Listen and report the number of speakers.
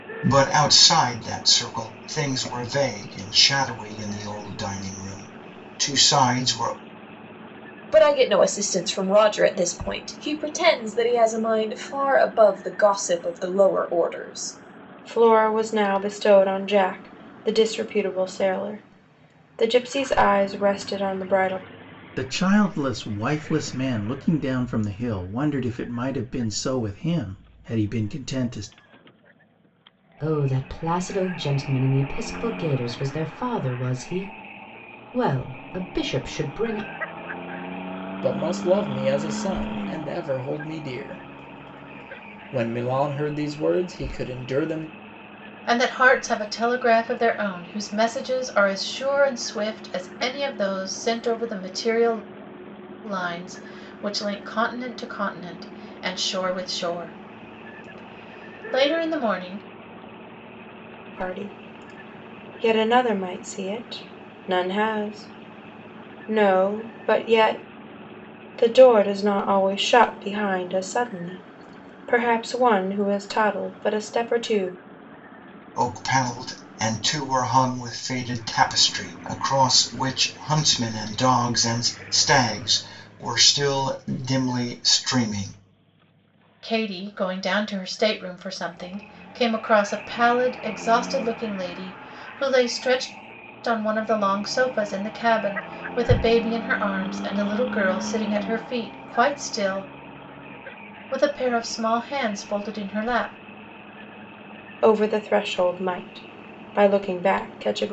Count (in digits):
7